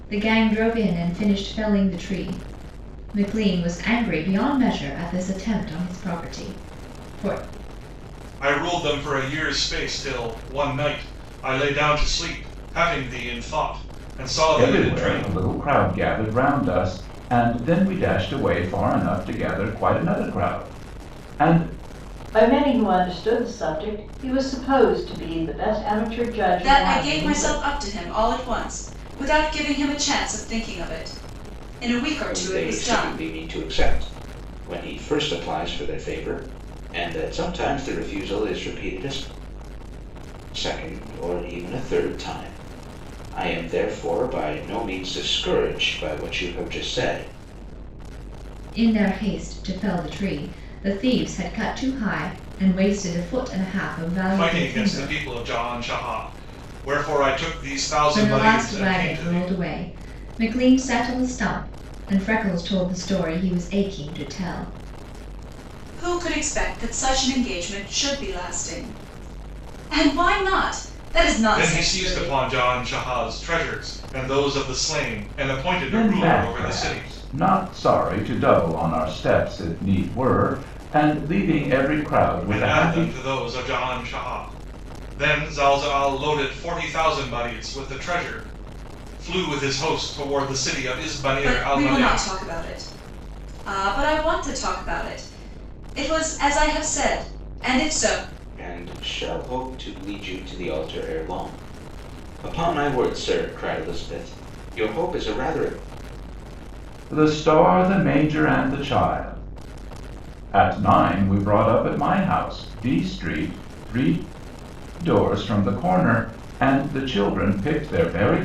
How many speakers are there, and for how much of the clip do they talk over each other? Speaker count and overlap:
six, about 8%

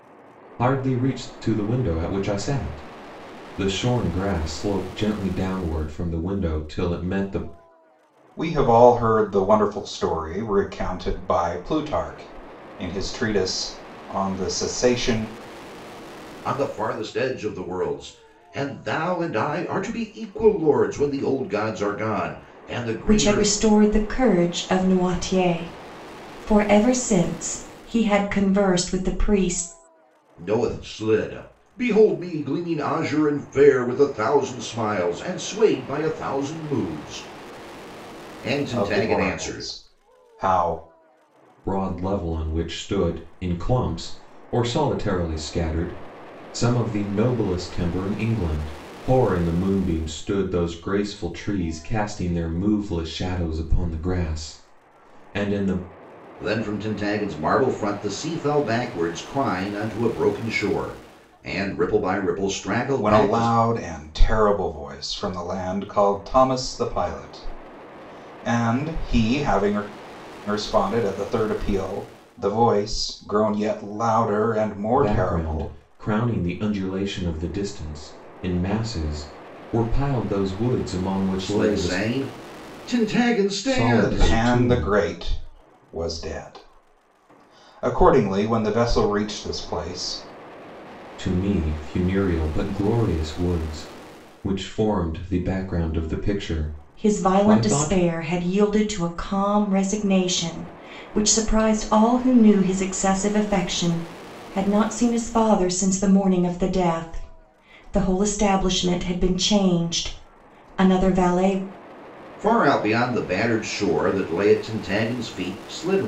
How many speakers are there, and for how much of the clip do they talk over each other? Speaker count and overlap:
four, about 5%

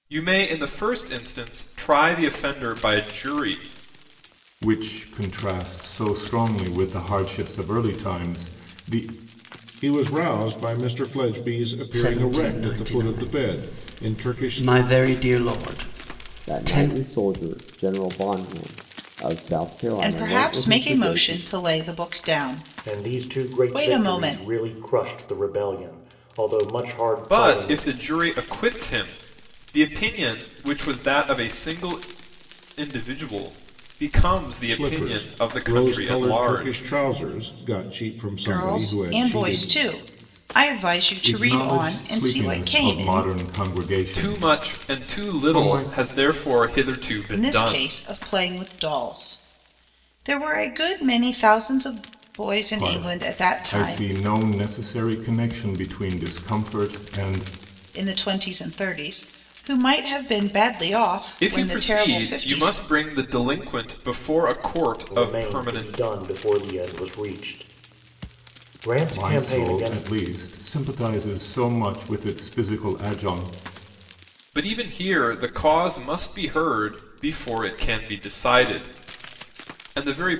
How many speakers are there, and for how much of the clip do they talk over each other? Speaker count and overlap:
seven, about 25%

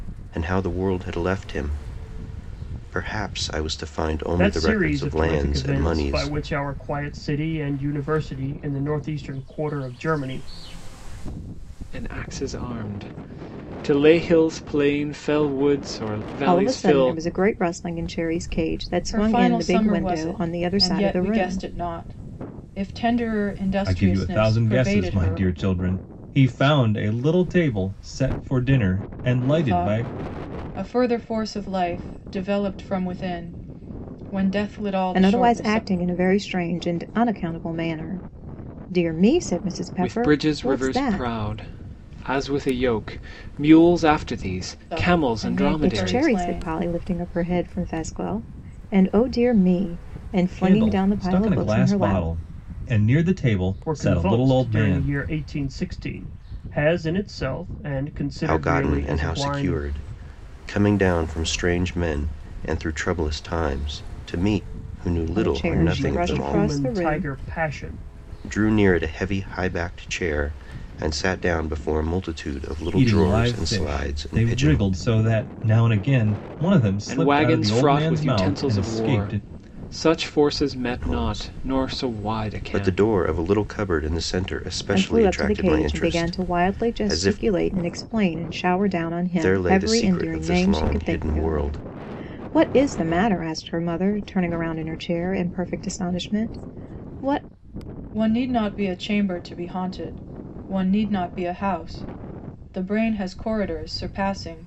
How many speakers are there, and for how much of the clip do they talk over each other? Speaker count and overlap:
six, about 28%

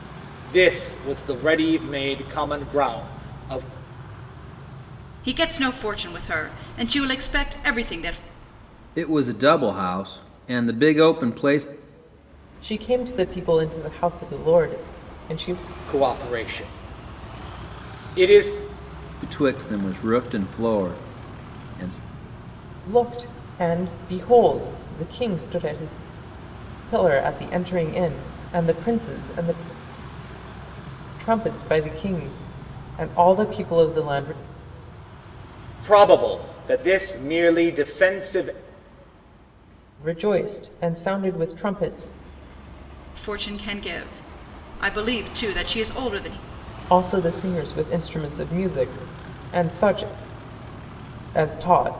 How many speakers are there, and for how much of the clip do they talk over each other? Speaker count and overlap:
four, no overlap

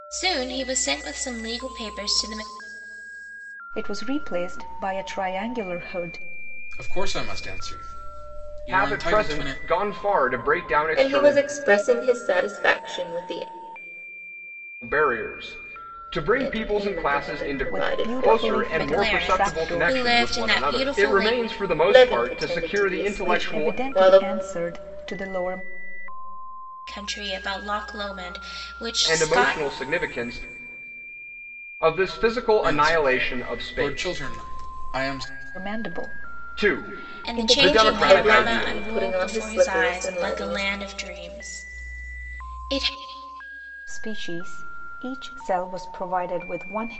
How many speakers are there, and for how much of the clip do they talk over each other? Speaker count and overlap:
five, about 33%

